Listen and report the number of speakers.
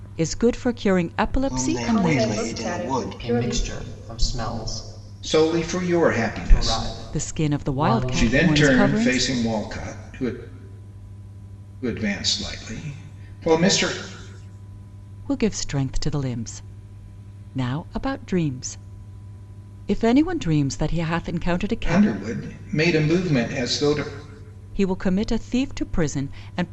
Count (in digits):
5